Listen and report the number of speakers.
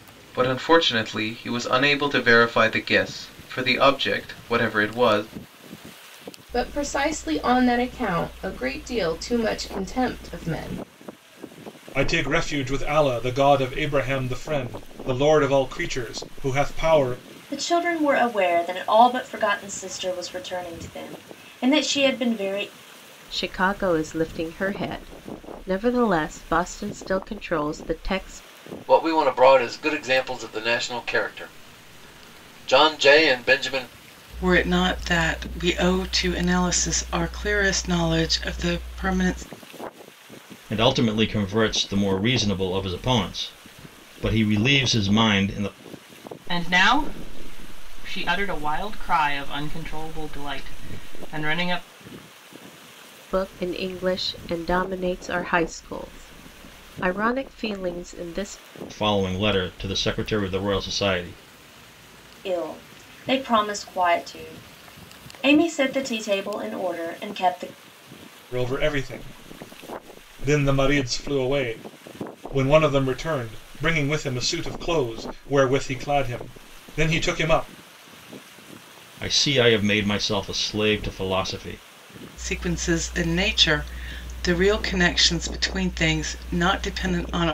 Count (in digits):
9